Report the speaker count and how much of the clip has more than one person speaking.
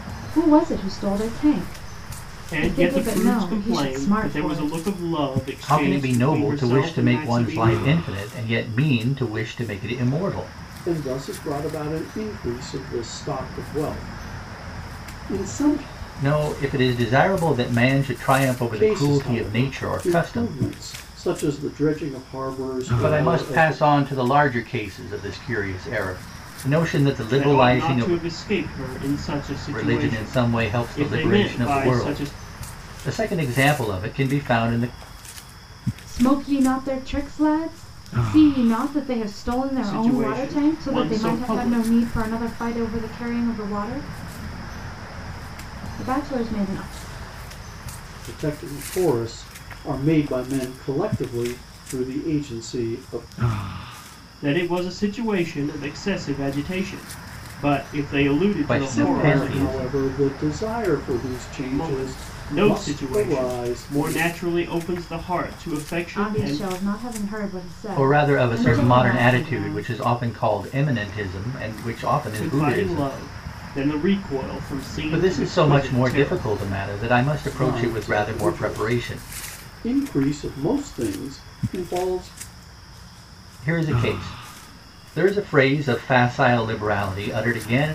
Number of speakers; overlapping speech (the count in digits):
4, about 27%